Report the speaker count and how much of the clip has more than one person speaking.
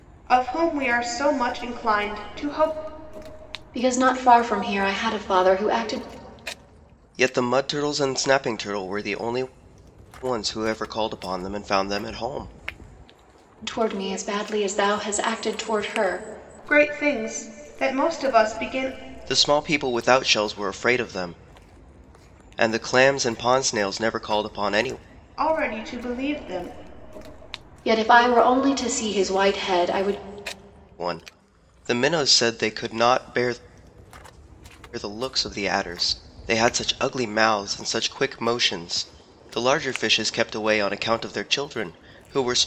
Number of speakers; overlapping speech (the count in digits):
3, no overlap